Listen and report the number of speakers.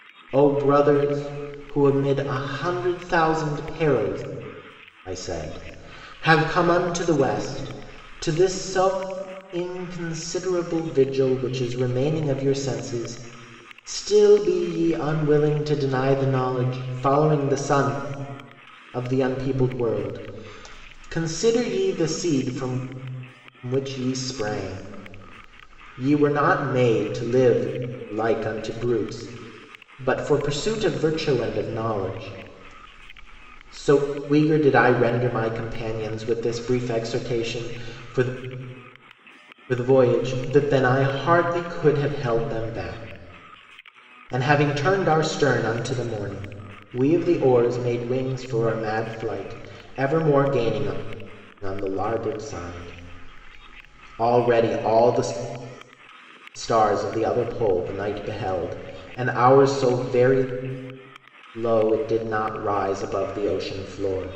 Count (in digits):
1